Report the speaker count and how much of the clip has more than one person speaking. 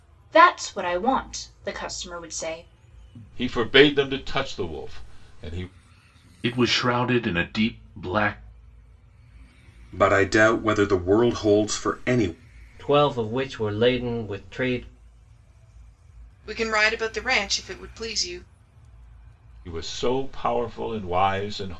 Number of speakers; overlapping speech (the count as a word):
six, no overlap